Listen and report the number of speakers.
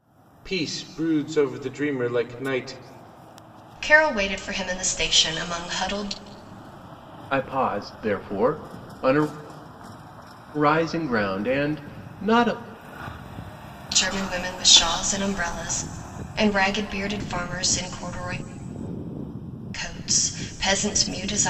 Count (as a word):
three